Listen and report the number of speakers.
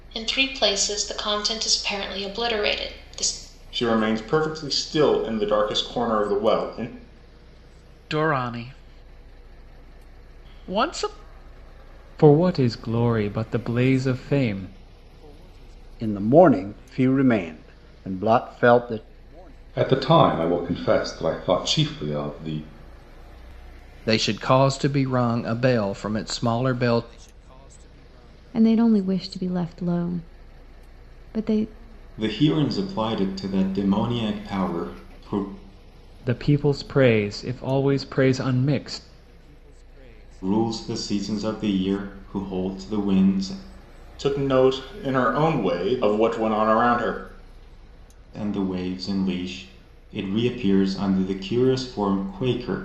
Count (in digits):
9